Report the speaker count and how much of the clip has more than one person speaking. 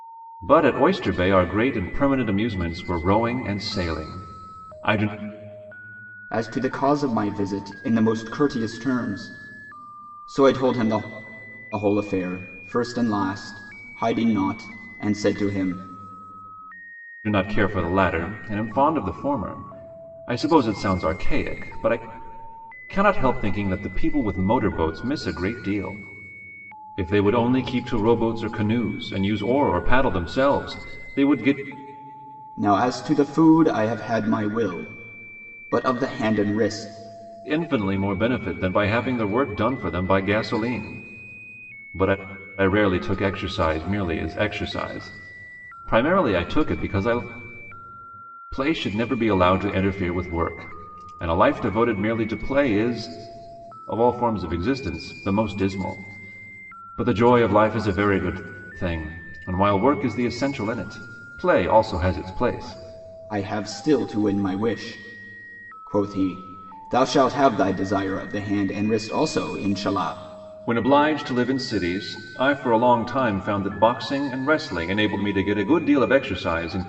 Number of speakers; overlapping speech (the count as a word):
two, no overlap